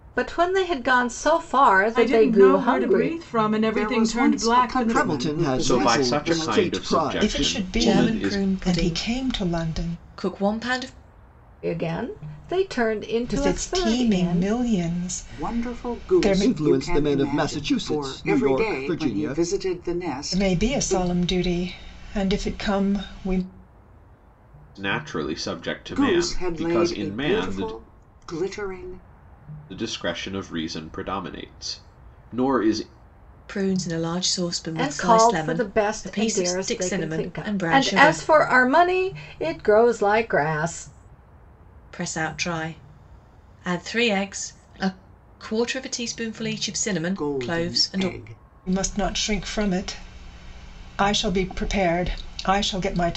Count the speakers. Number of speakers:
7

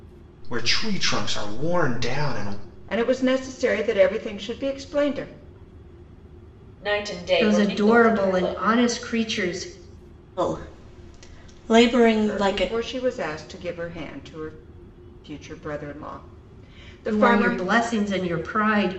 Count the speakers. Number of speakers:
5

